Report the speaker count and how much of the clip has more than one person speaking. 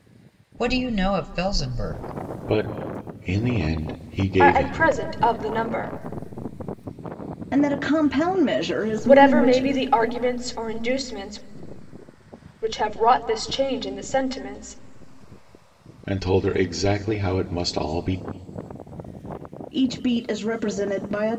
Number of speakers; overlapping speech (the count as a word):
four, about 6%